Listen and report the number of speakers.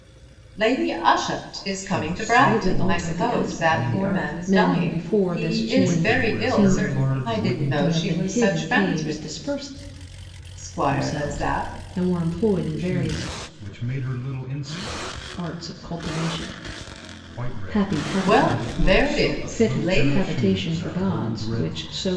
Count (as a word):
three